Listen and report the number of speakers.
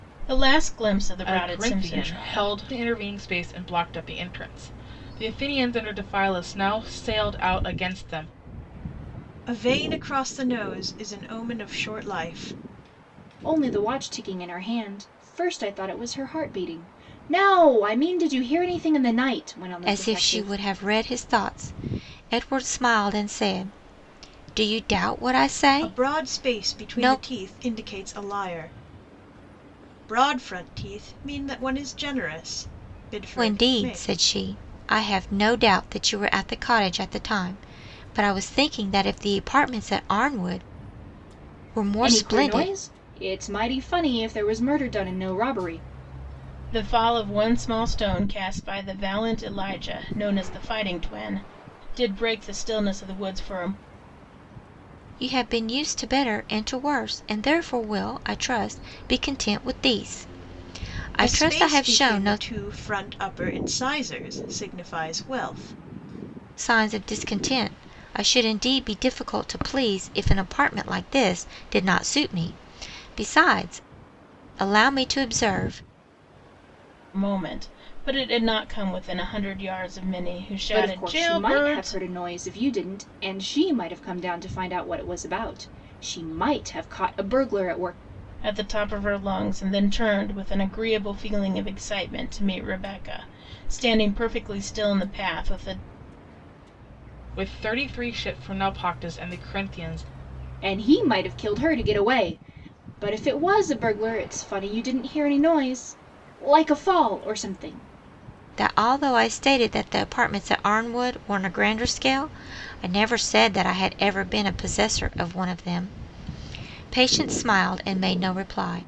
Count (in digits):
5